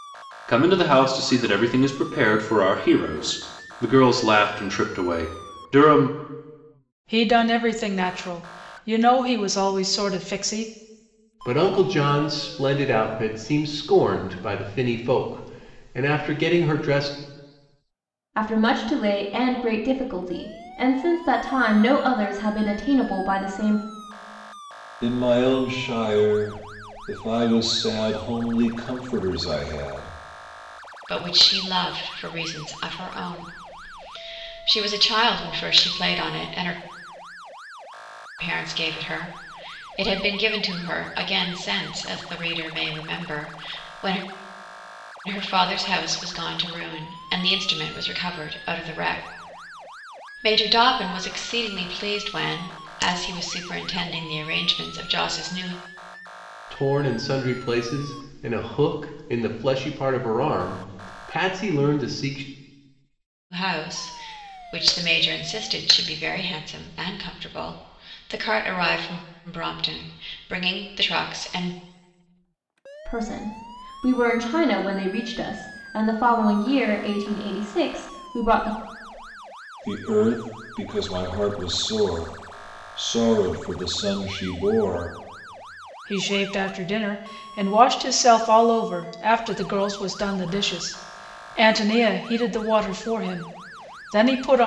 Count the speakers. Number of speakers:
6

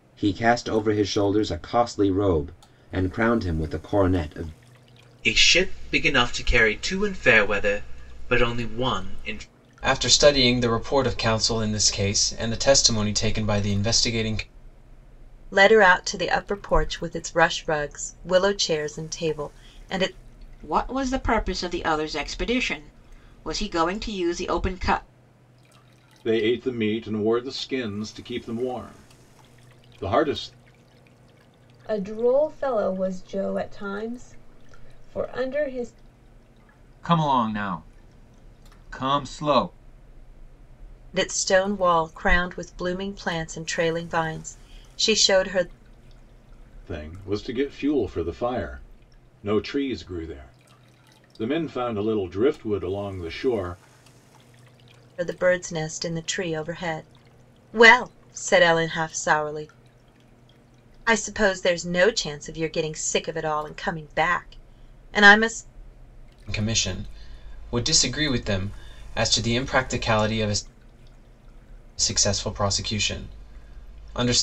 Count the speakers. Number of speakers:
8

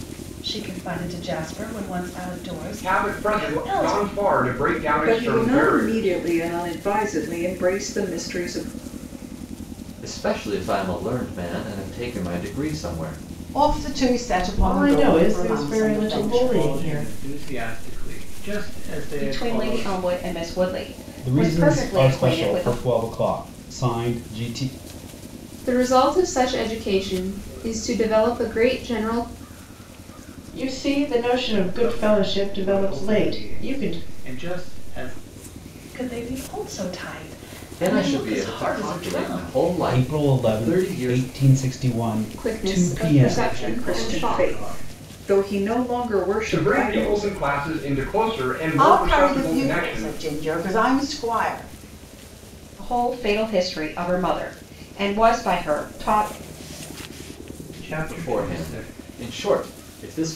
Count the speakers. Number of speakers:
10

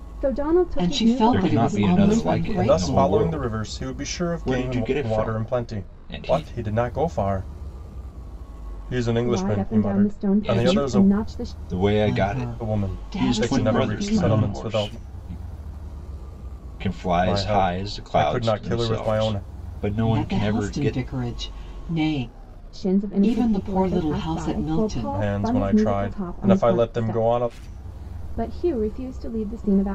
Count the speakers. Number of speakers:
4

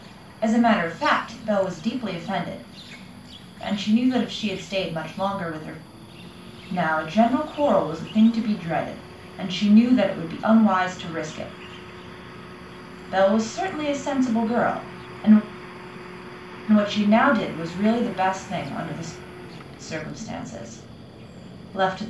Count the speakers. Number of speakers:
1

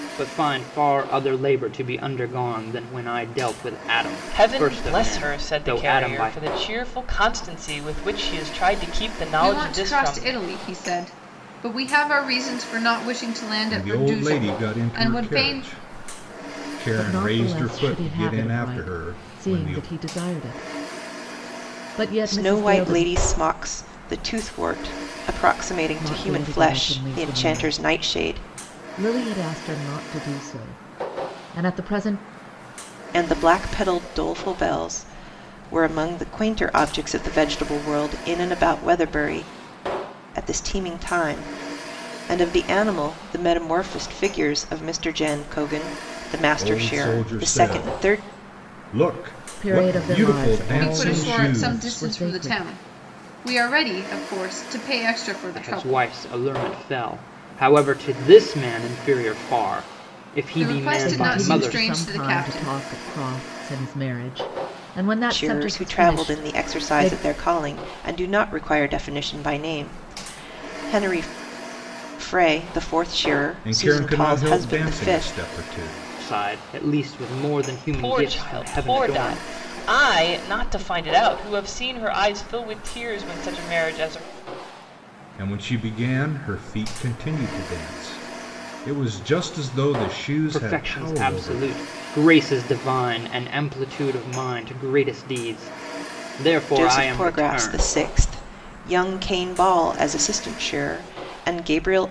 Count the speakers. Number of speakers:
6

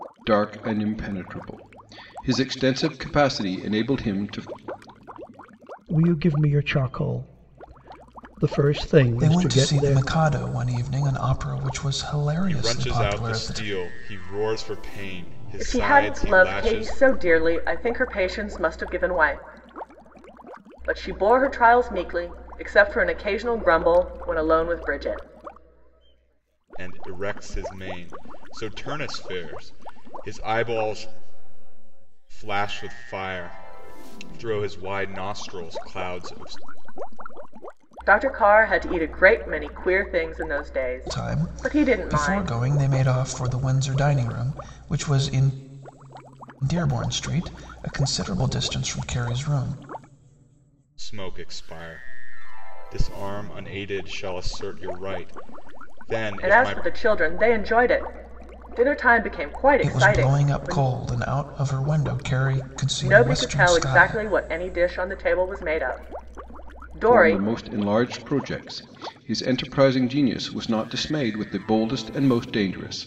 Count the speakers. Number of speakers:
5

